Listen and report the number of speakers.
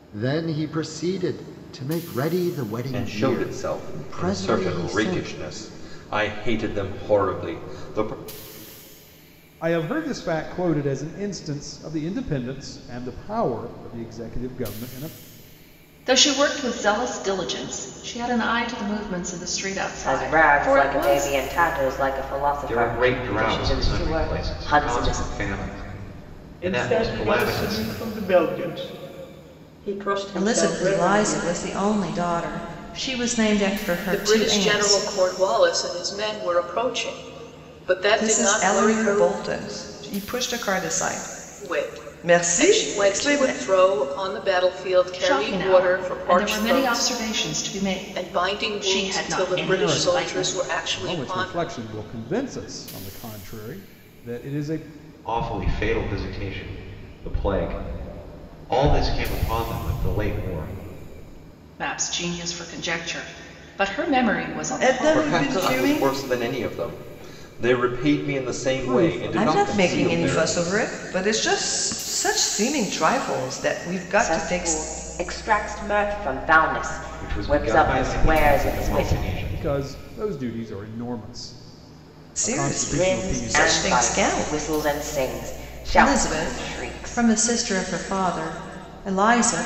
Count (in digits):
10